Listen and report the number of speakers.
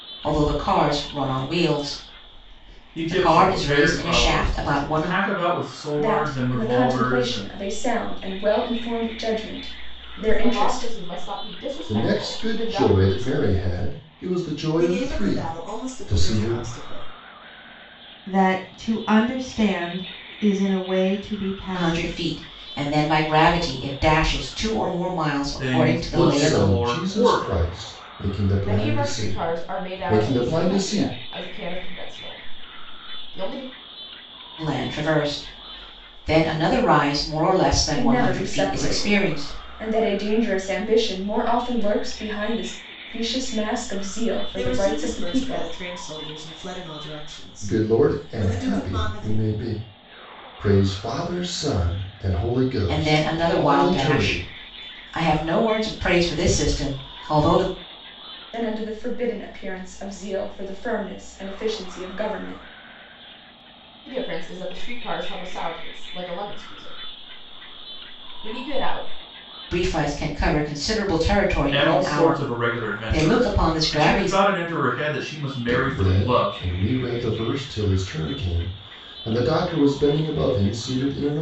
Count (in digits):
7